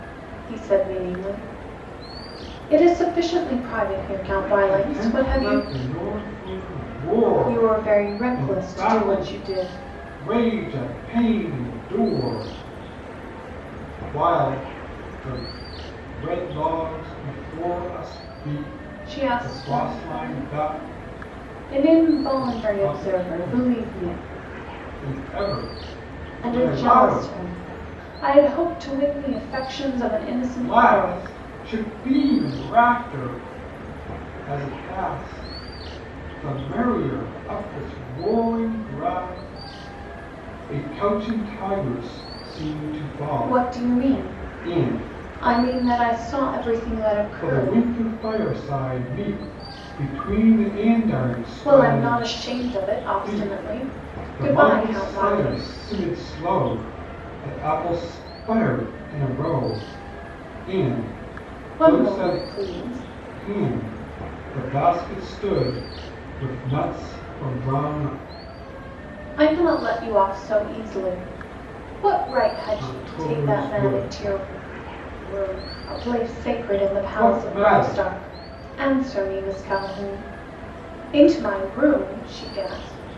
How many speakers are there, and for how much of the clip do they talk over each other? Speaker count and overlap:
two, about 23%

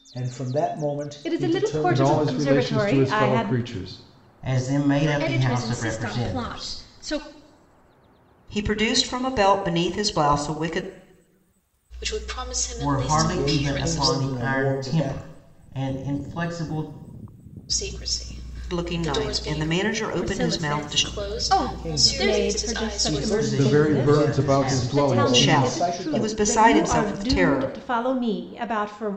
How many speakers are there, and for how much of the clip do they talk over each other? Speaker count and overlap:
seven, about 53%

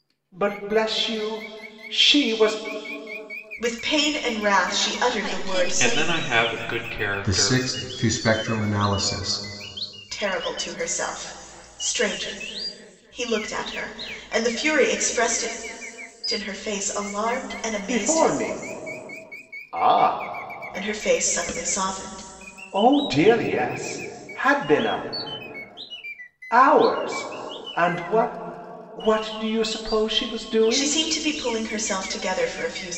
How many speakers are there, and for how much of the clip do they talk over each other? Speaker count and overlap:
five, about 7%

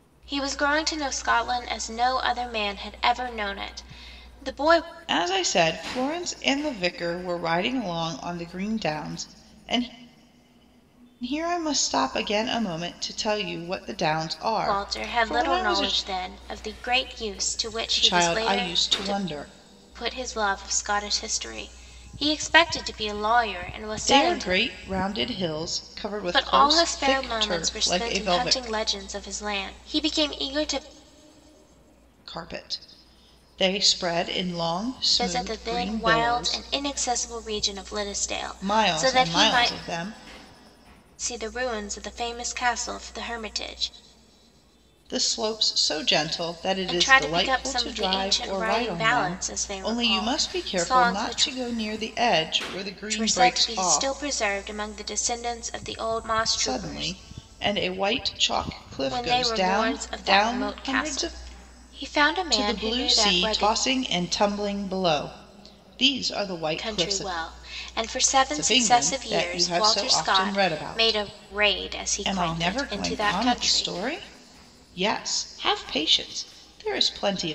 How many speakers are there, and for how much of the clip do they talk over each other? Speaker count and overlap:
two, about 31%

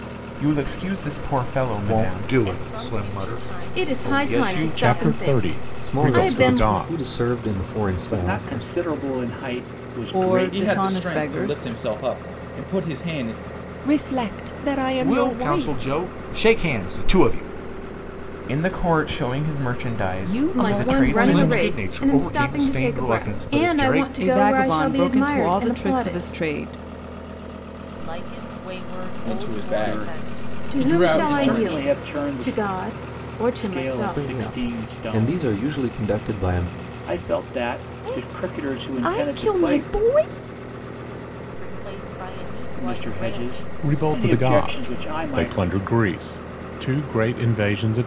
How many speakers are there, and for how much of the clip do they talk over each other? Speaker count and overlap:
ten, about 50%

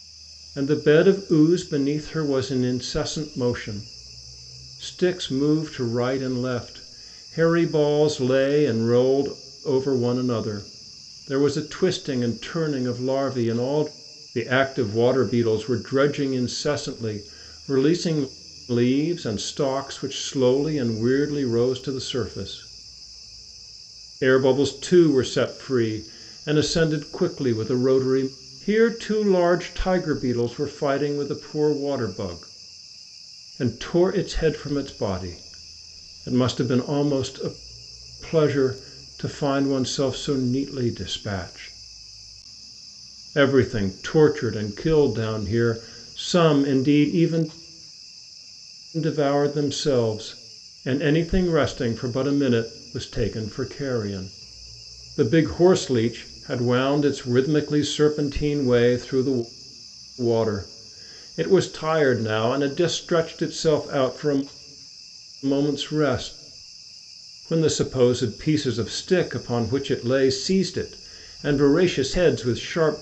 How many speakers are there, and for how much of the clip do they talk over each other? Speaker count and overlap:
one, no overlap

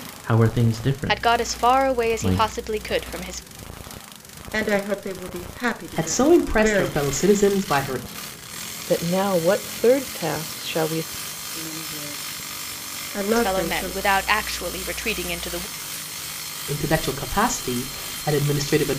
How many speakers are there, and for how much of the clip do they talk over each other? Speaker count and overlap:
five, about 16%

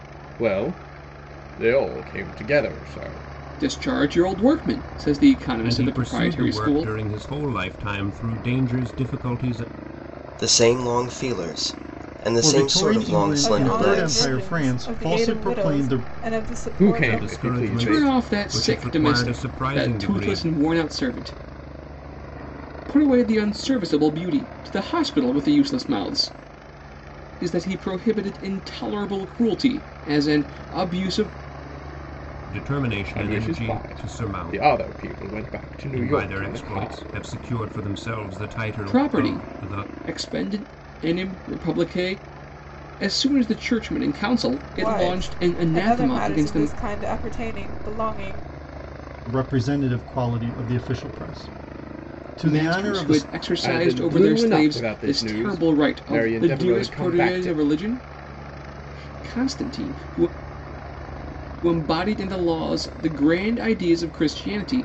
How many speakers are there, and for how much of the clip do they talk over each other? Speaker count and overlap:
six, about 30%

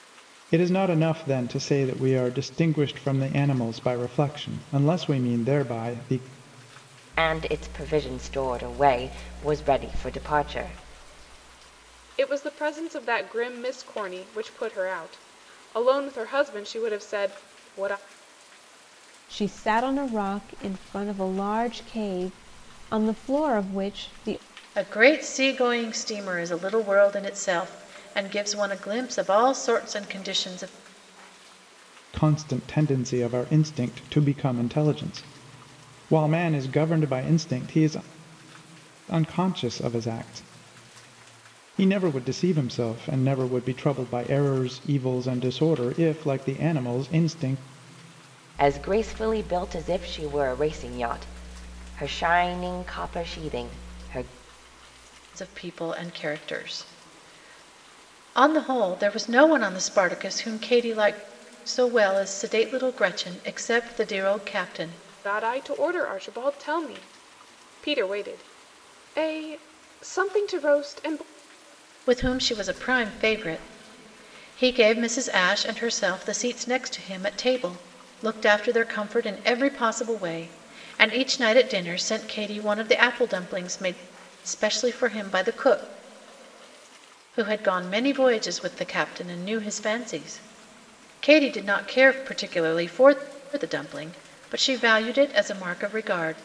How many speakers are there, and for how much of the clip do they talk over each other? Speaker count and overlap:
five, no overlap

